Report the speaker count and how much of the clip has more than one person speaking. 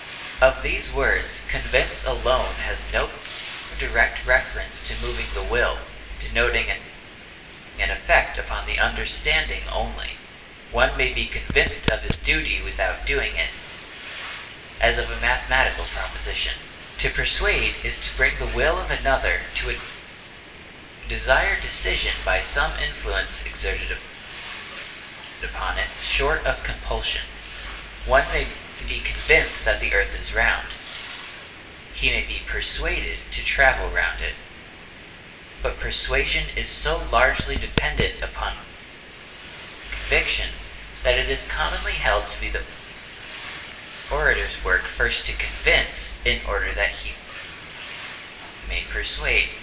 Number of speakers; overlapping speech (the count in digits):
1, no overlap